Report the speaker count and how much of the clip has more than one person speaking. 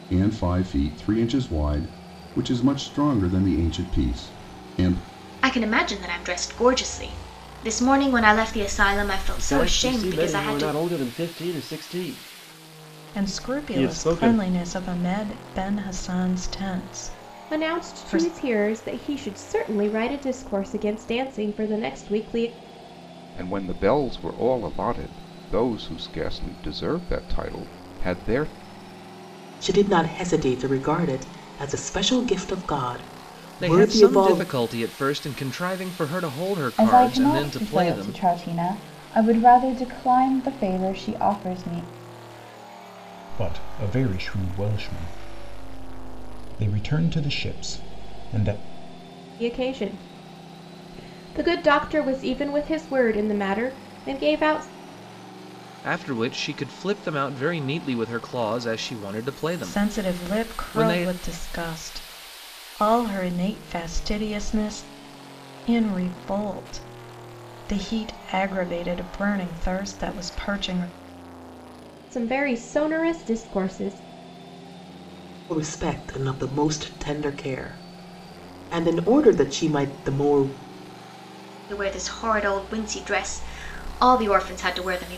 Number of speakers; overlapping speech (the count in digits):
10, about 9%